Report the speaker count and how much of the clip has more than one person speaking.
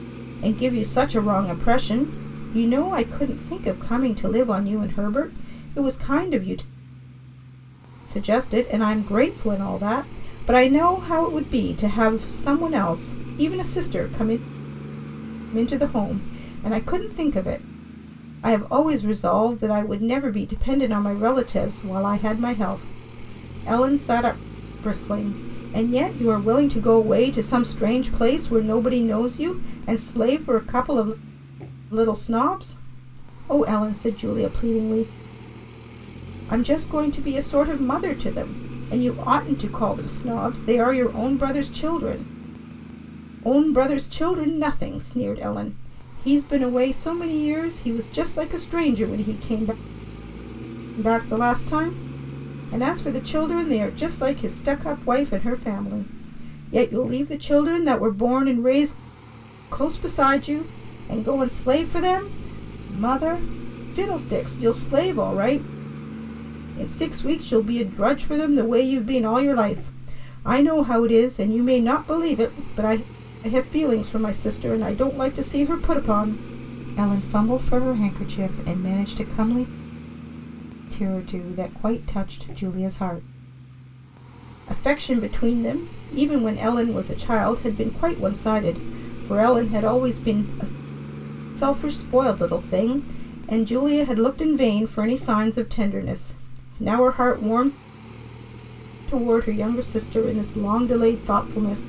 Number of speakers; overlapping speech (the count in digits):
1, no overlap